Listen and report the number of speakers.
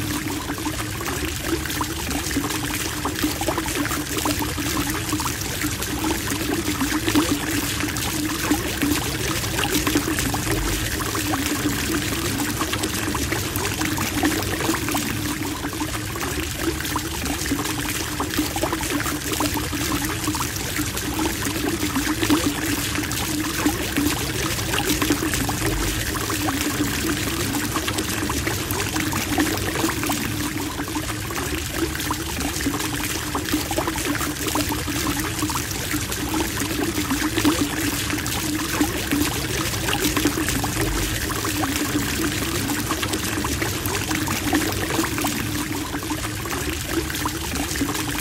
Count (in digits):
0